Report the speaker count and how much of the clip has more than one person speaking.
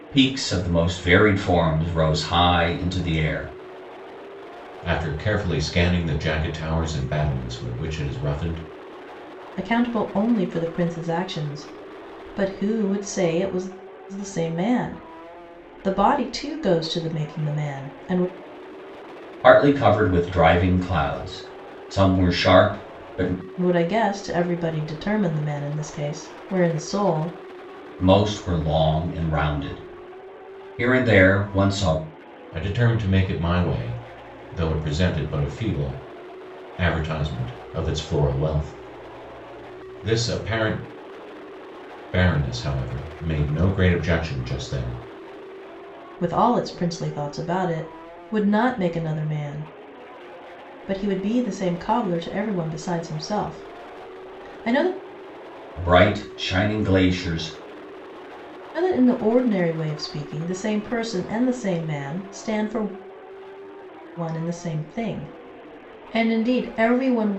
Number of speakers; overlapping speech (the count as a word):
three, no overlap